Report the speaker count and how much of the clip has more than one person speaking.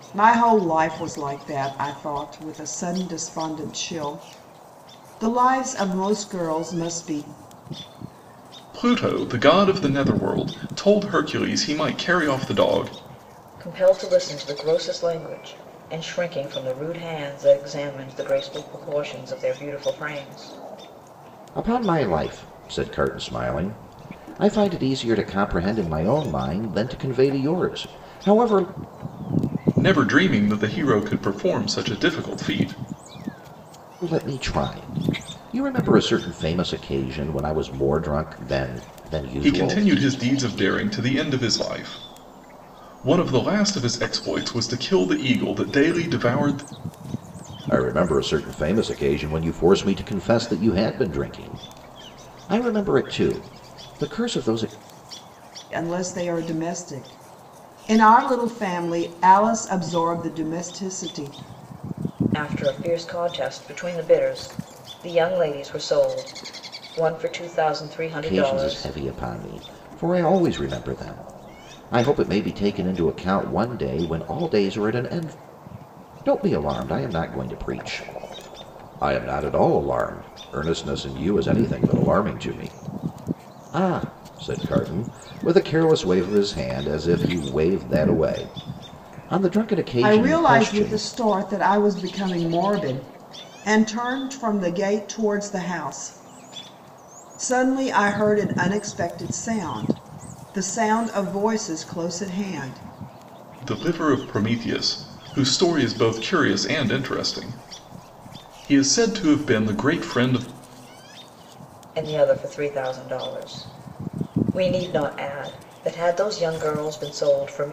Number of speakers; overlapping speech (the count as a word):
four, about 2%